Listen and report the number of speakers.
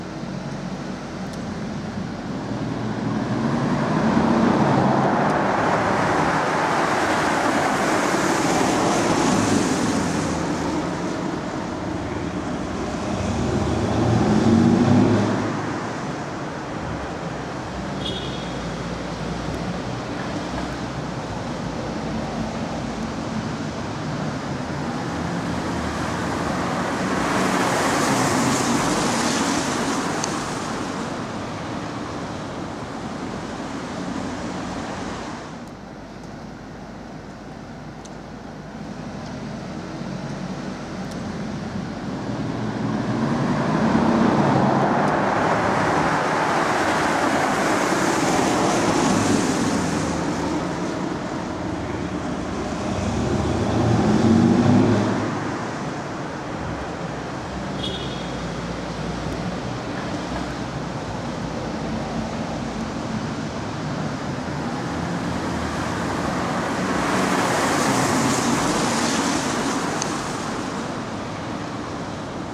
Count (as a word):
zero